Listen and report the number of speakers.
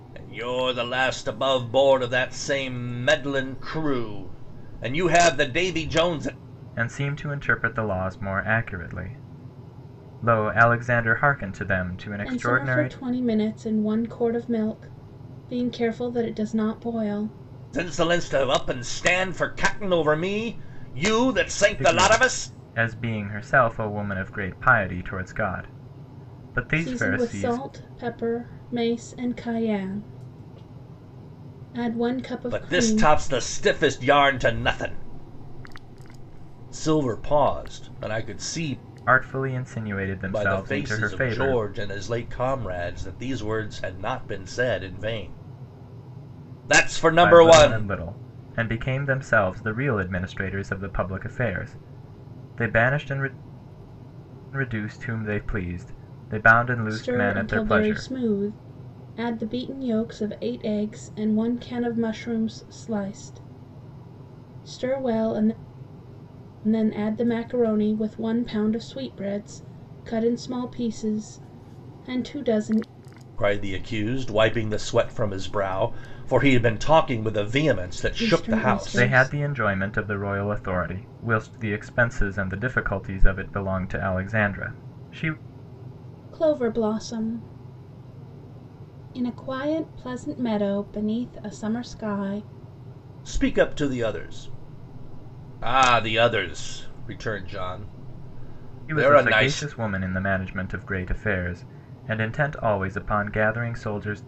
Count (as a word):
three